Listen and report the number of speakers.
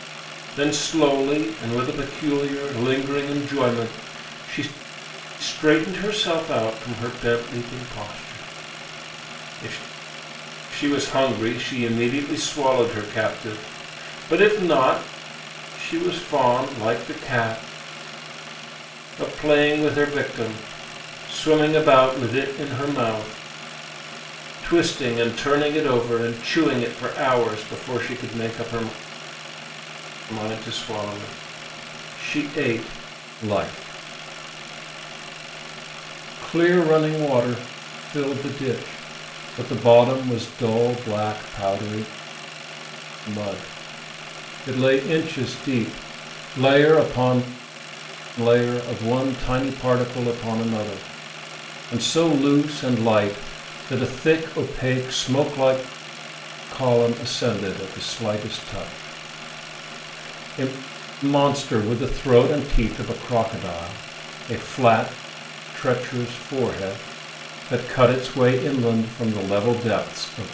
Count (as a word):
one